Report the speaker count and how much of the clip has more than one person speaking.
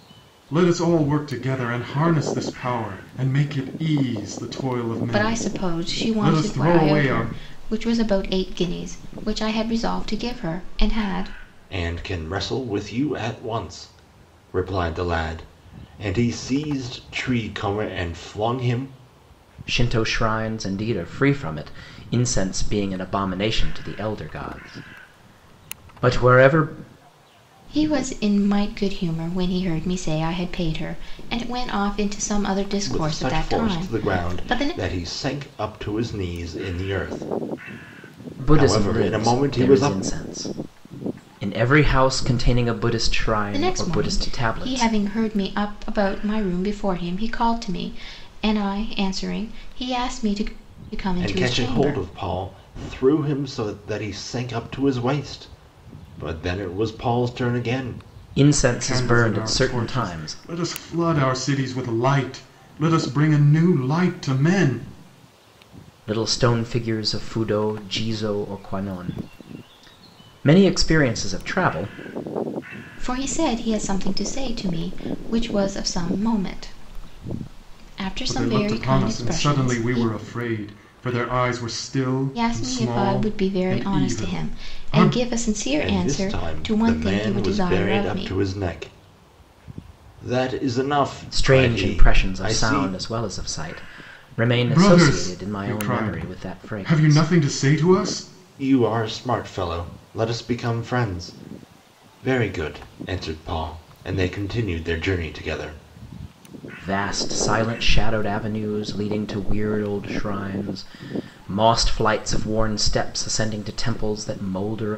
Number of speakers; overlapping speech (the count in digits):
4, about 18%